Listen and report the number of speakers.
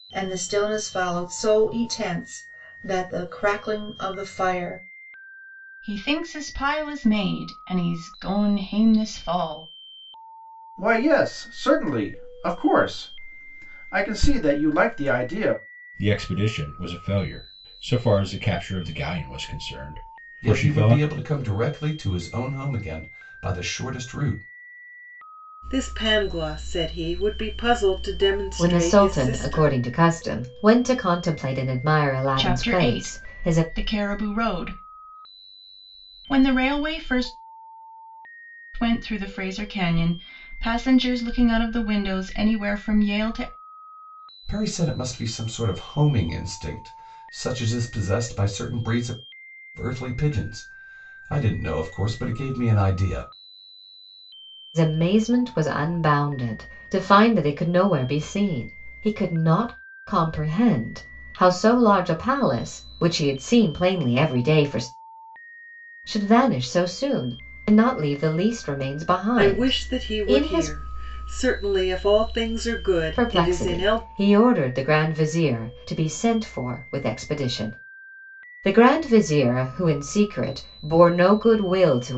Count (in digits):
7